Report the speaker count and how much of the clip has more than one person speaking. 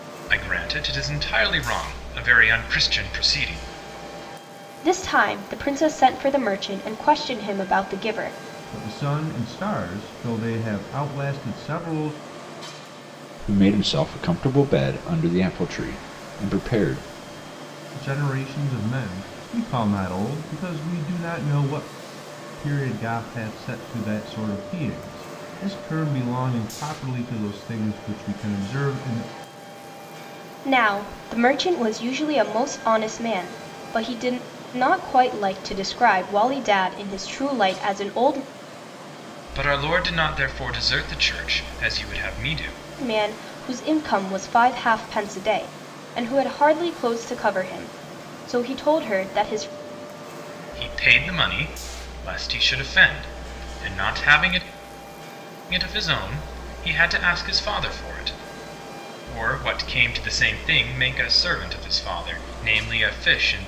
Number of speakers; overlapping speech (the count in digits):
4, no overlap